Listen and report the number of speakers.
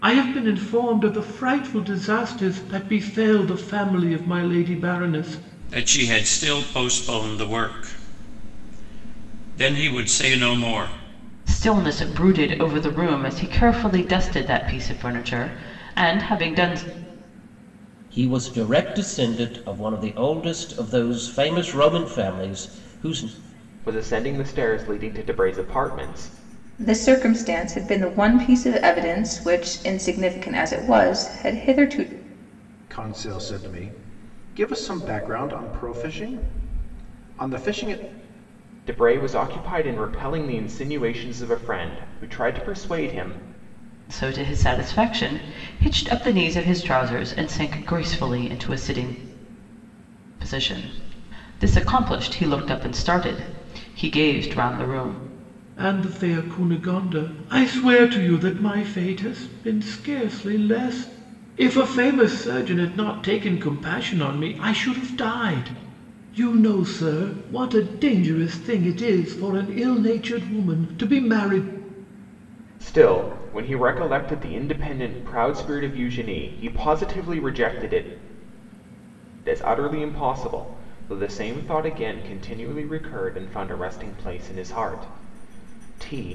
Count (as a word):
seven